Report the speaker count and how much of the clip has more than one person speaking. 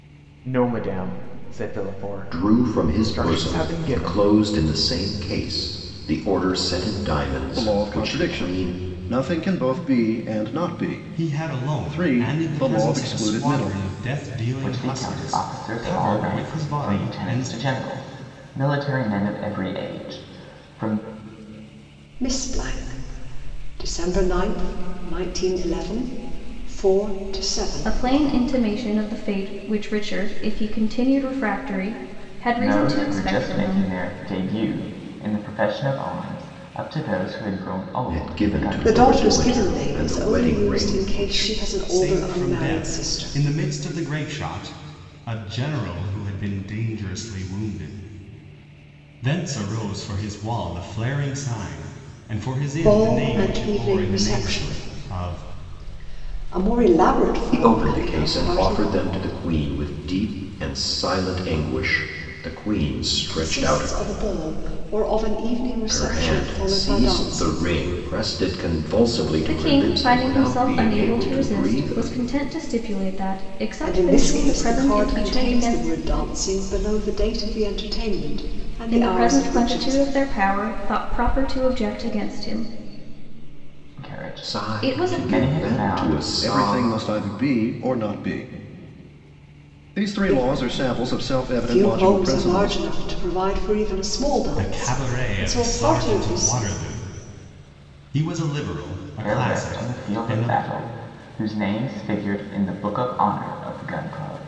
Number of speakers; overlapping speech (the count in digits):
7, about 36%